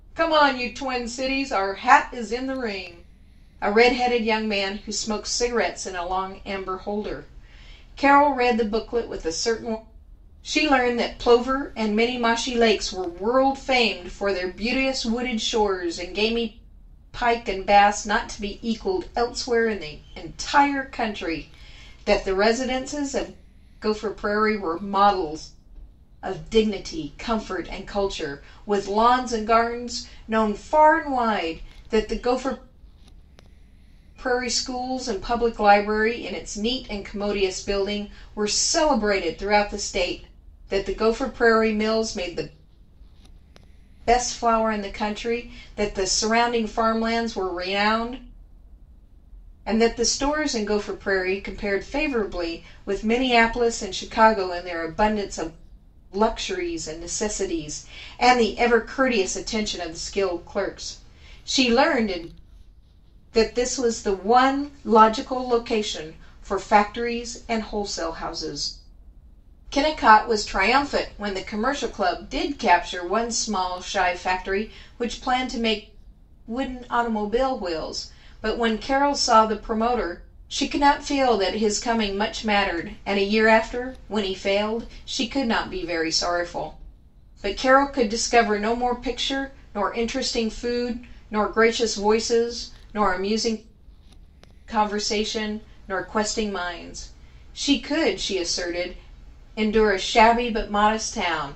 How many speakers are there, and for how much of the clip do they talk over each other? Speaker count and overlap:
1, no overlap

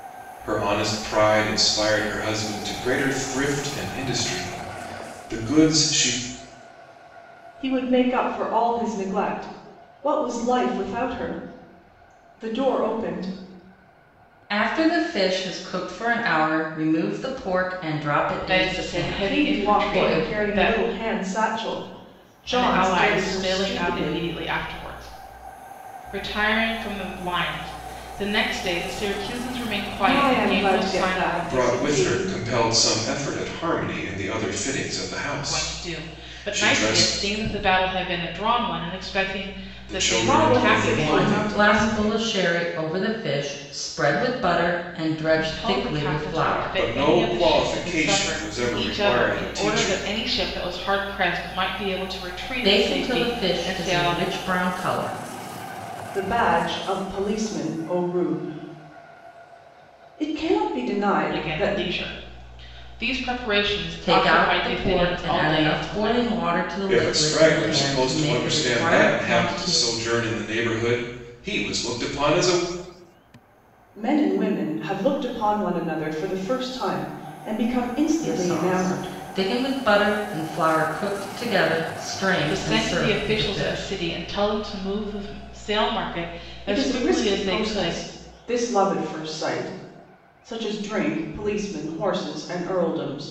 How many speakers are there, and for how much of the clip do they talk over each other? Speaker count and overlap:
4, about 29%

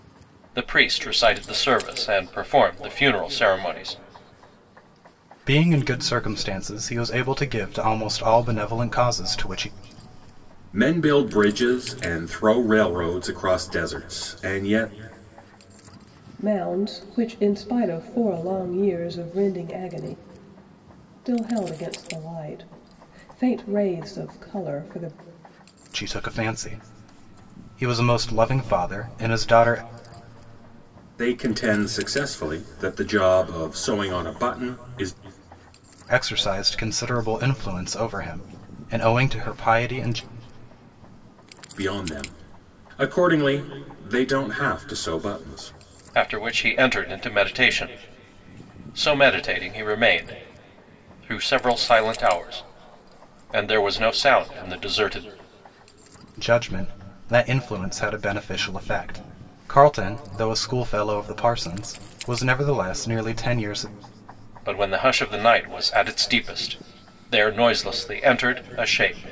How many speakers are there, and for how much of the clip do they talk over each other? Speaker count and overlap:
4, no overlap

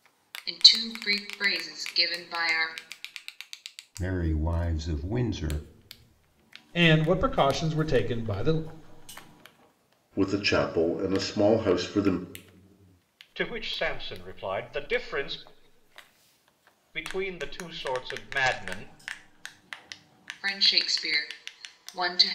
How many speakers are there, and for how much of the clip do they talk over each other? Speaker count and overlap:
5, no overlap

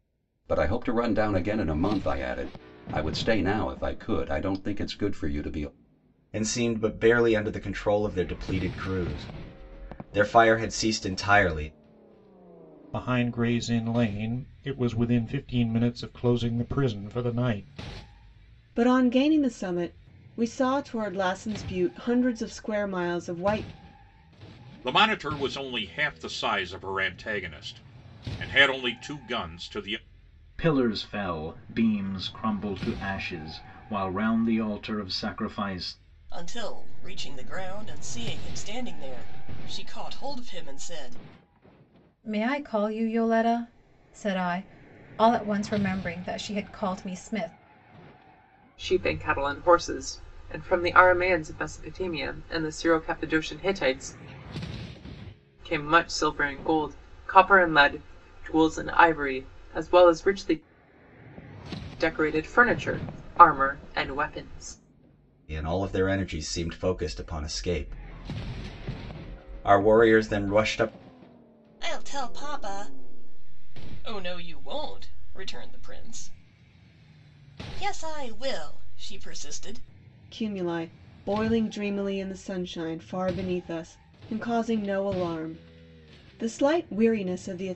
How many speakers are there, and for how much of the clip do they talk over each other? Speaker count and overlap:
9, no overlap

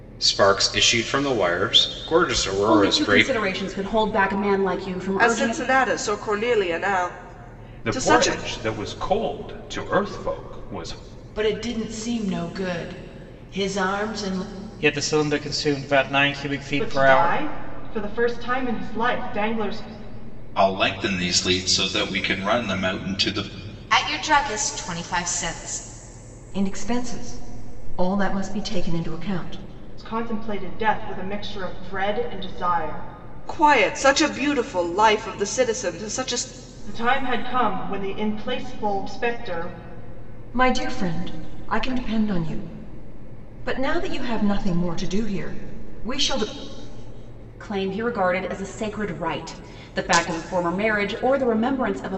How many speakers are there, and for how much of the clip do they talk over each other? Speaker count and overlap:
10, about 5%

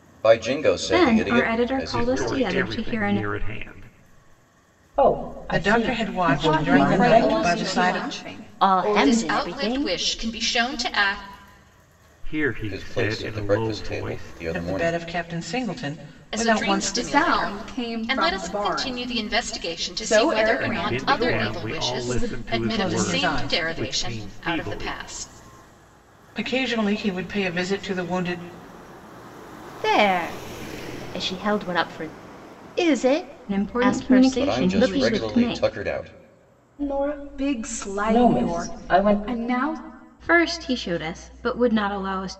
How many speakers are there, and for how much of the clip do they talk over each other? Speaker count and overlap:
9, about 50%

